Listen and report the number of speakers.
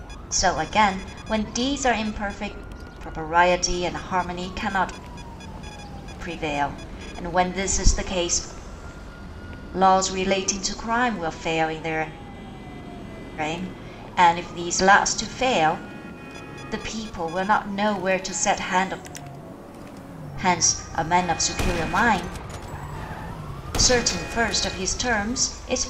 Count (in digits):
1